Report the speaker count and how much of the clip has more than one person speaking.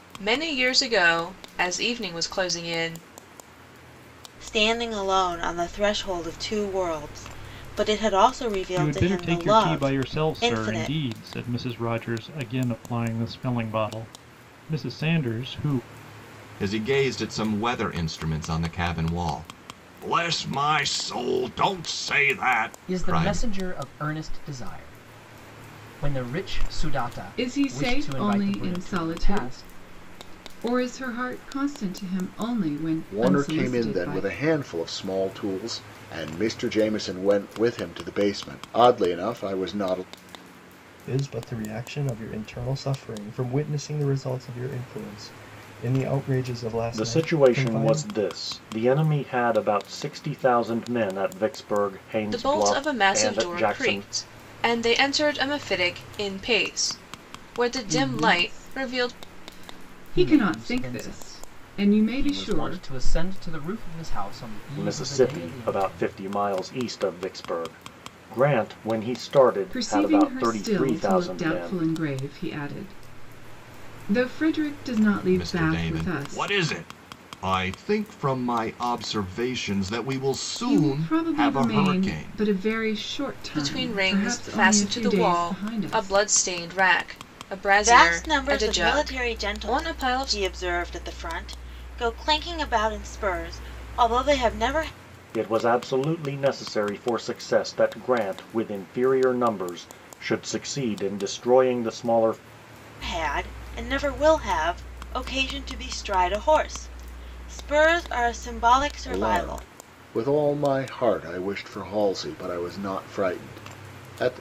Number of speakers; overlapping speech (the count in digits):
9, about 23%